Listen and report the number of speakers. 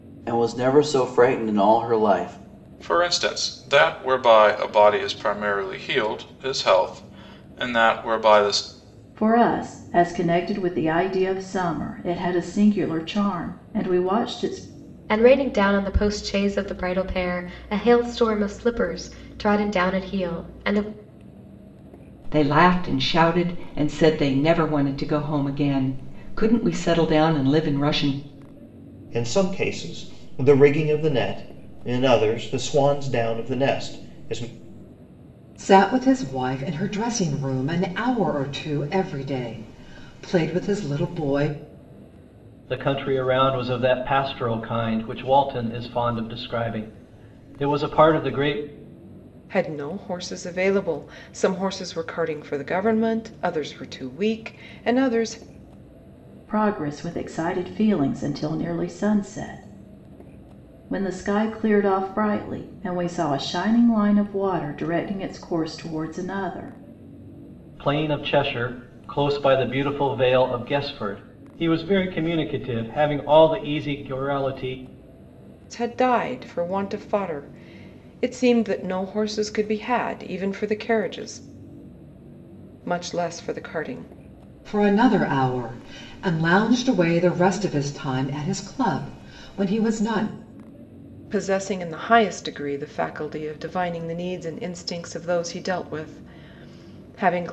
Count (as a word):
nine